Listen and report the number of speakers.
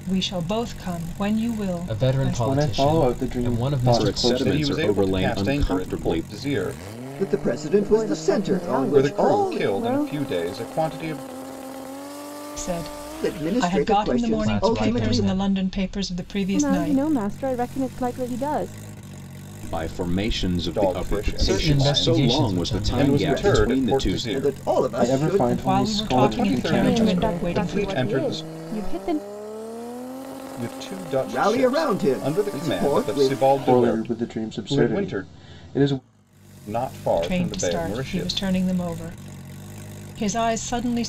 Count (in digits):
7